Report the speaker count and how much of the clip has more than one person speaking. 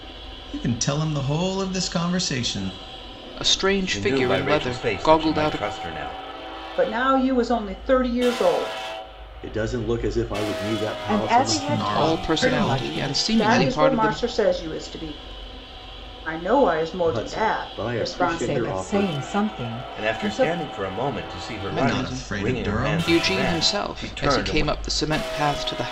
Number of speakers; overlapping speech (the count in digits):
6, about 41%